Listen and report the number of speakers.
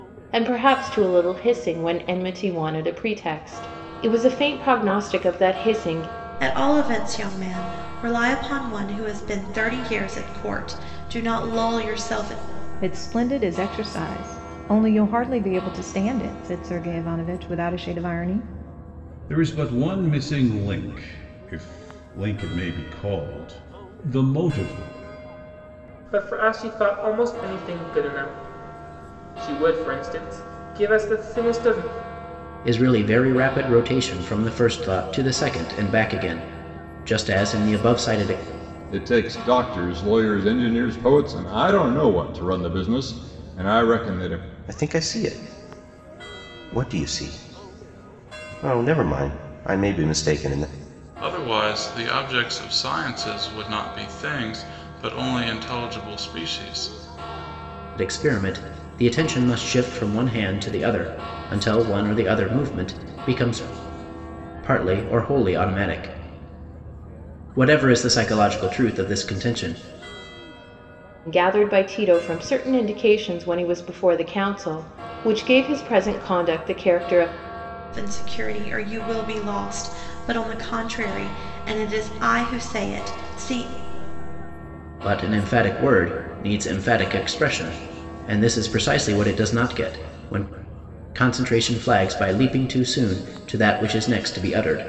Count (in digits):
9